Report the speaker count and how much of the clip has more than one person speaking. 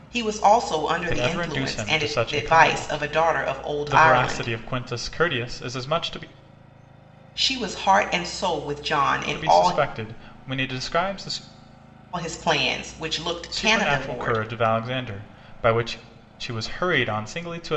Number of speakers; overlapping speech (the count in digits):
2, about 22%